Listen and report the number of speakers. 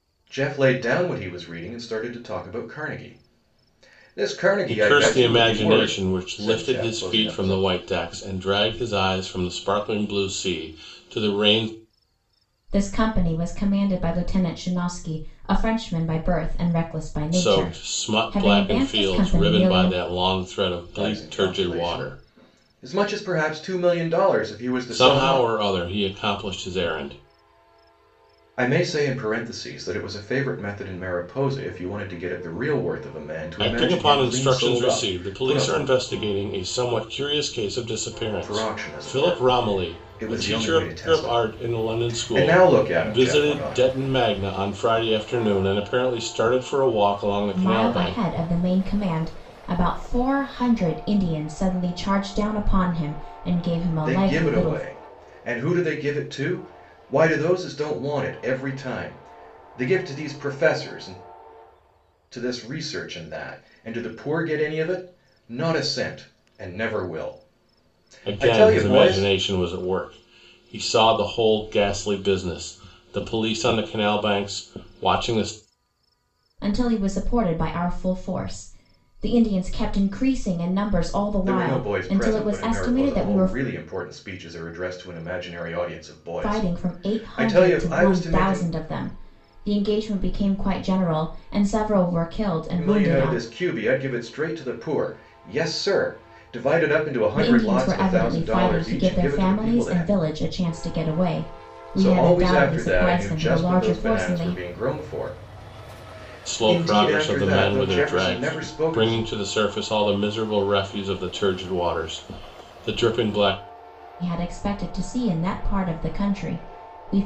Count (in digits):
3